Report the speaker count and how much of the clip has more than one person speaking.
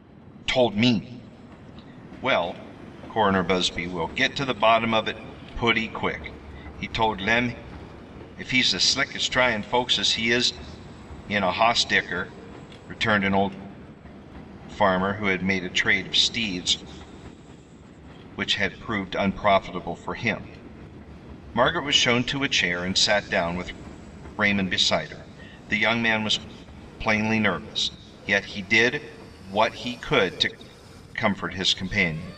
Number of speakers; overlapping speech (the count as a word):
one, no overlap